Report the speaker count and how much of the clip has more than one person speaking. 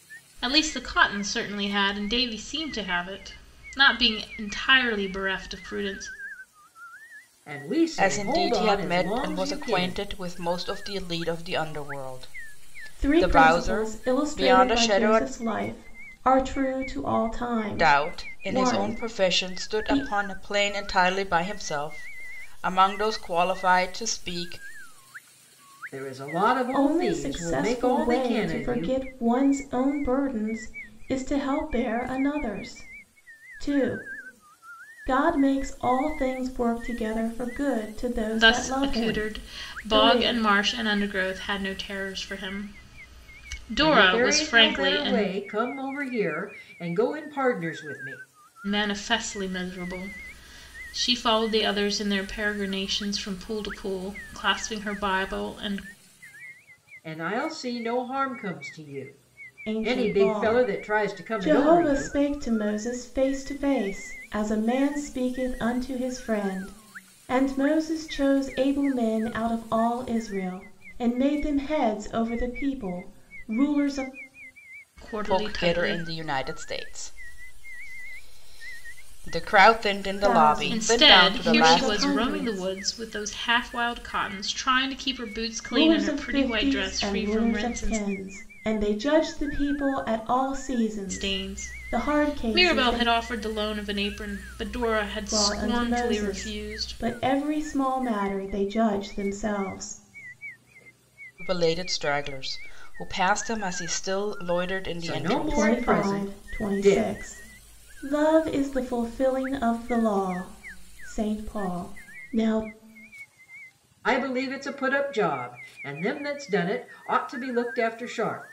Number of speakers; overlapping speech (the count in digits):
4, about 23%